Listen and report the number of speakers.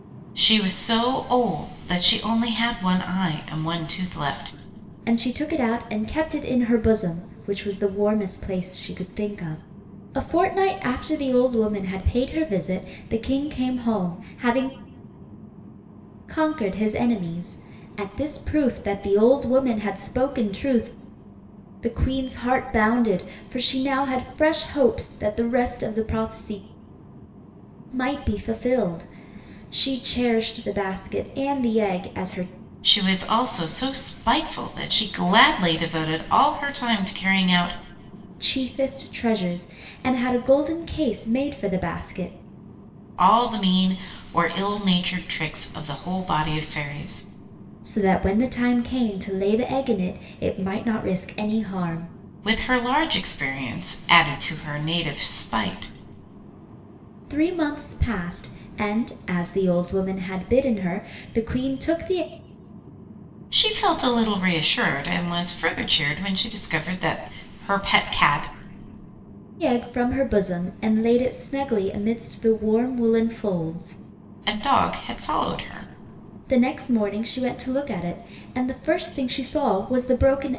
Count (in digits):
2